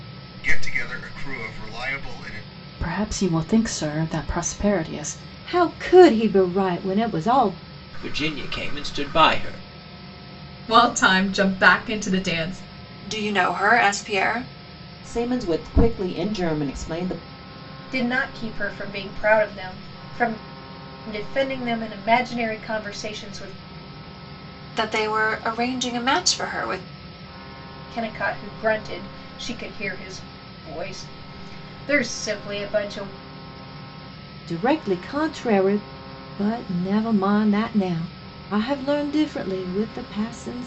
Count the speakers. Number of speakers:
8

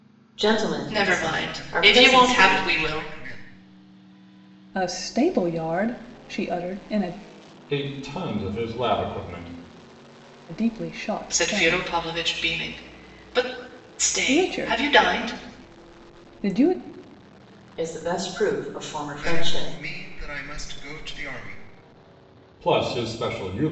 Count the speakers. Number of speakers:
5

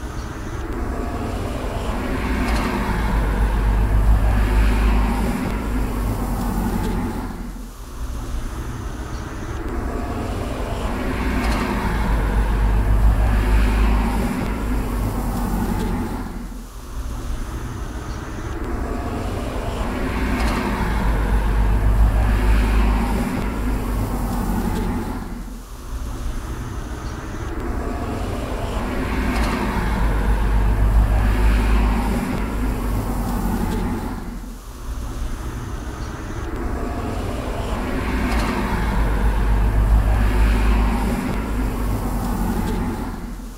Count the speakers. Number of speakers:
0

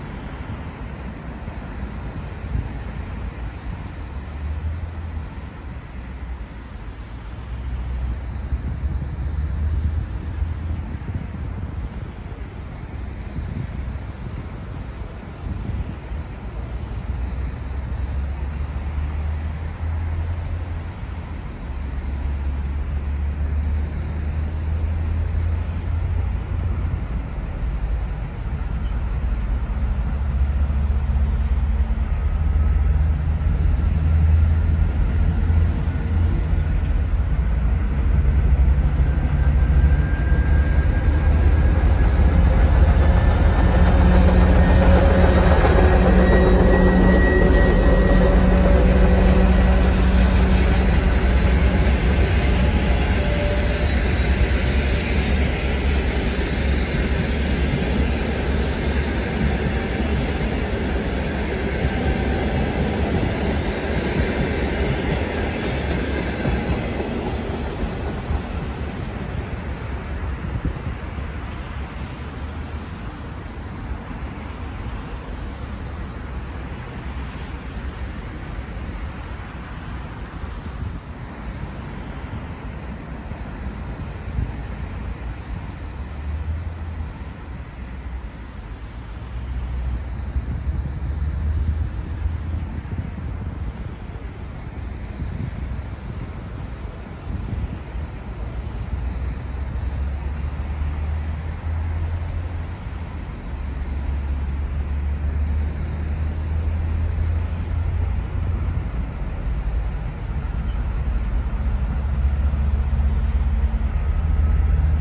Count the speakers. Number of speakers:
0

